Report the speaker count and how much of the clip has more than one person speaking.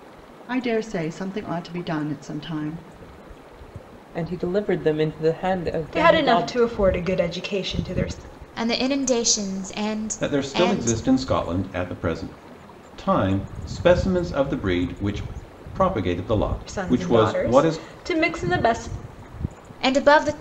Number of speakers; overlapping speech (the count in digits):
5, about 14%